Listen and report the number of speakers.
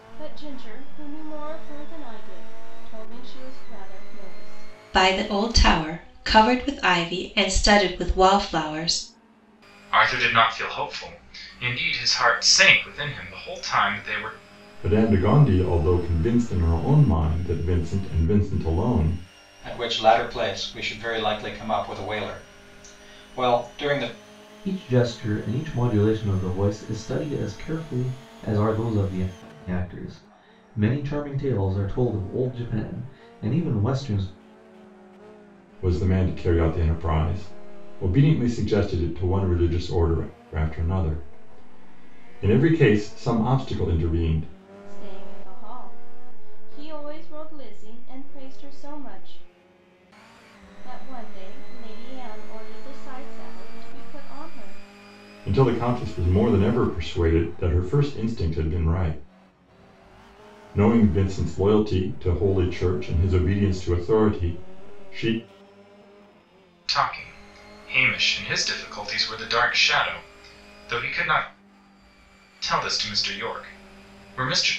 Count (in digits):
6